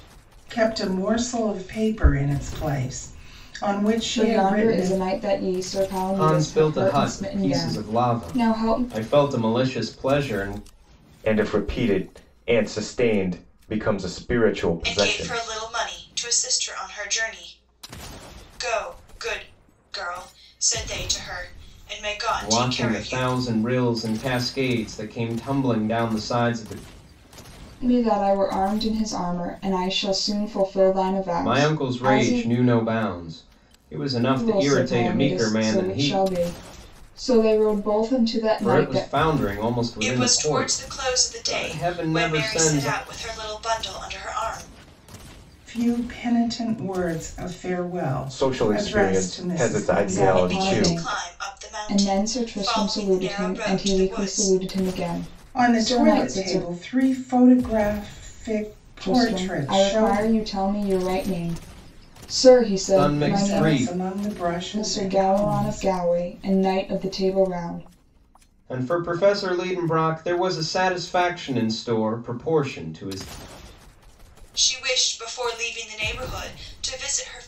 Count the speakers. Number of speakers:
5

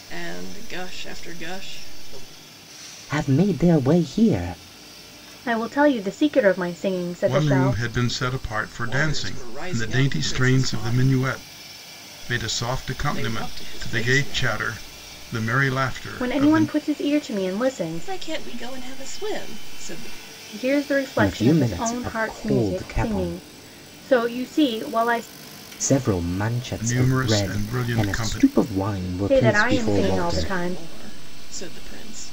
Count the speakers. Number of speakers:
4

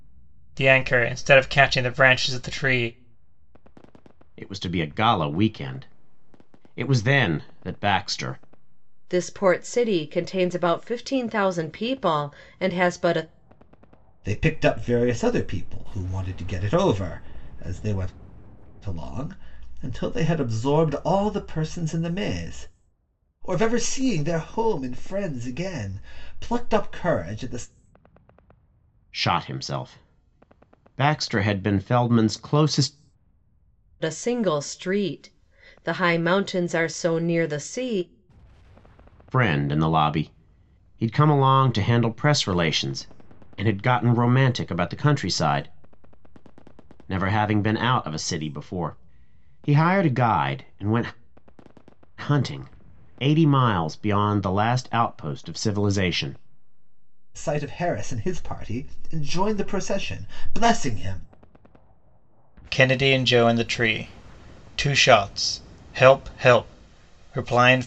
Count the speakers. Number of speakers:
4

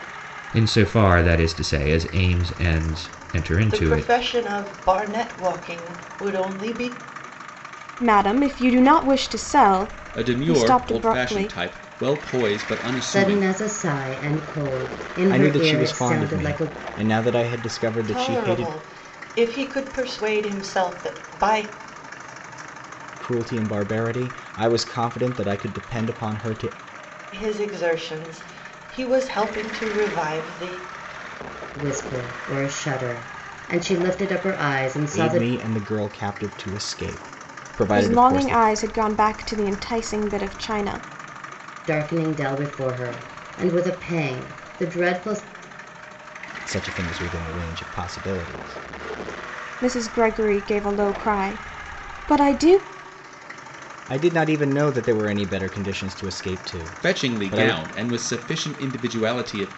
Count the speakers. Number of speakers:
6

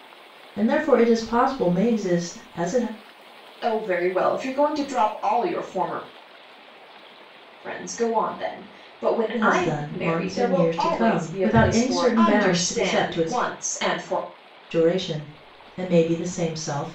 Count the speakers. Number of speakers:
2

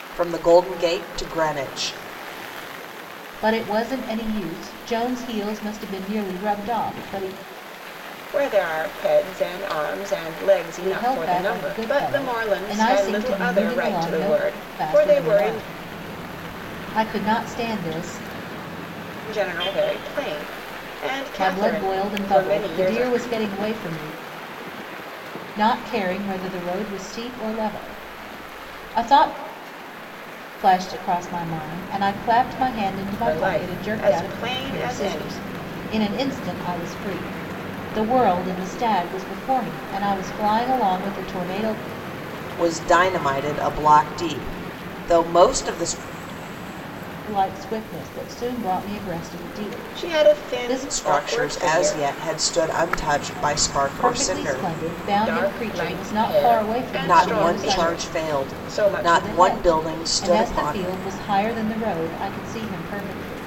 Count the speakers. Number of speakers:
3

